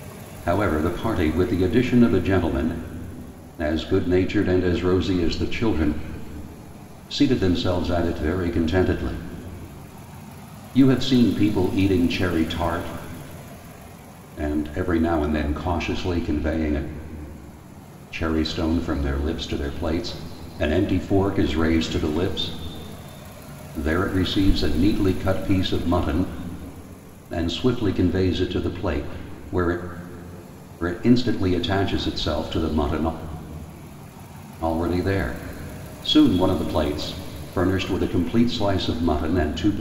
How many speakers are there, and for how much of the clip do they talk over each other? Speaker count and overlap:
one, no overlap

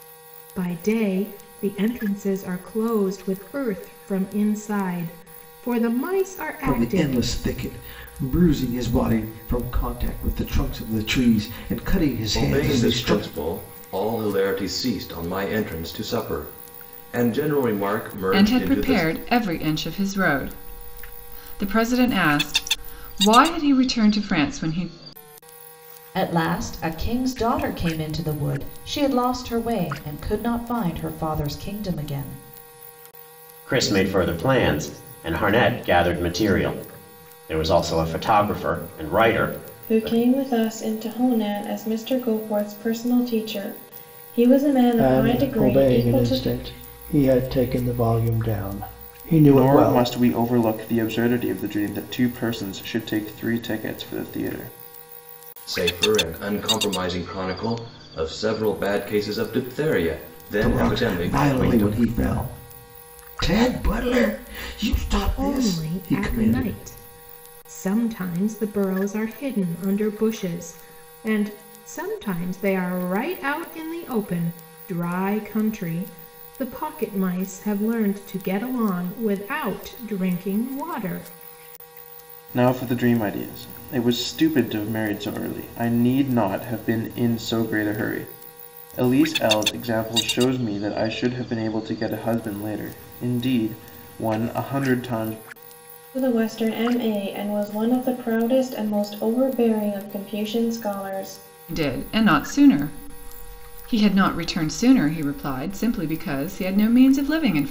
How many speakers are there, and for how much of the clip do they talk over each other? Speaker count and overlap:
nine, about 7%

